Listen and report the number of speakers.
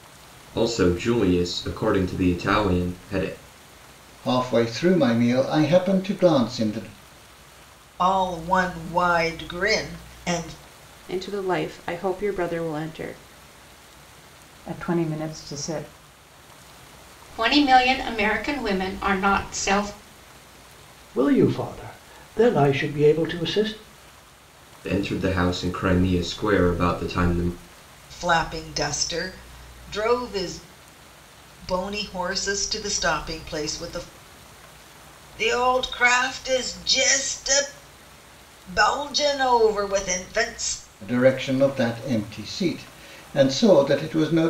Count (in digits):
7